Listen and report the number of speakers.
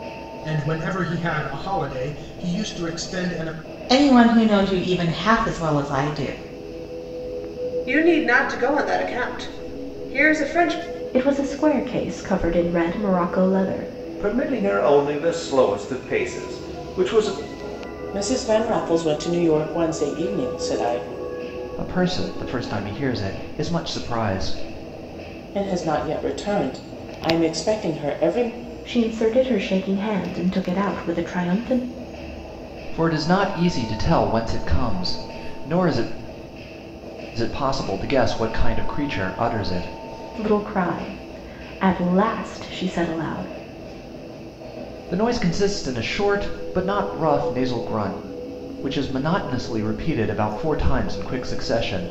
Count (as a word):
seven